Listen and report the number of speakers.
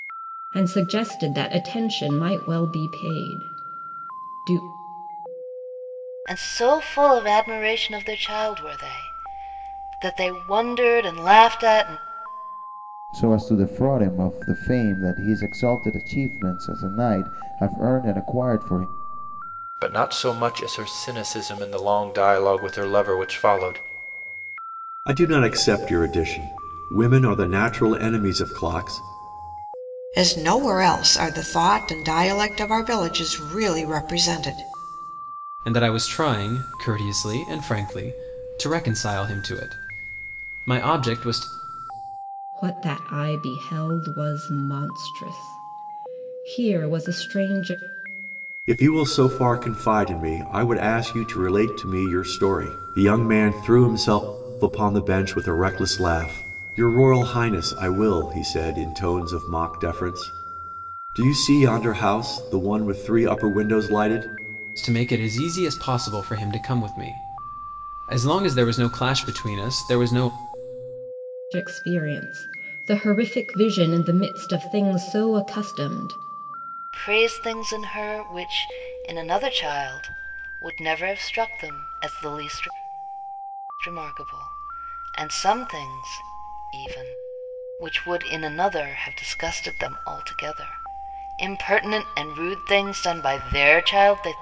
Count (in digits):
7